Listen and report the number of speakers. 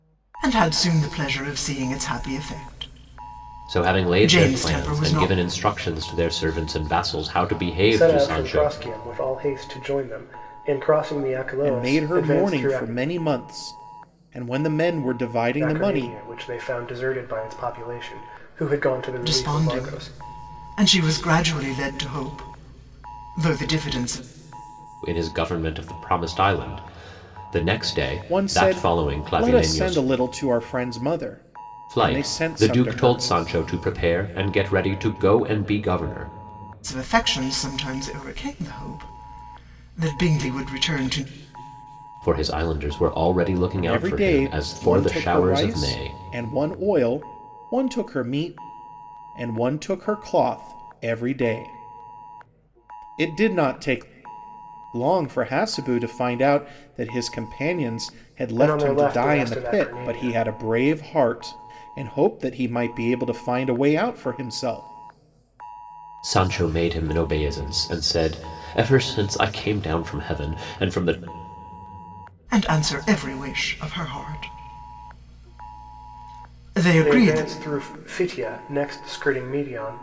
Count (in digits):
4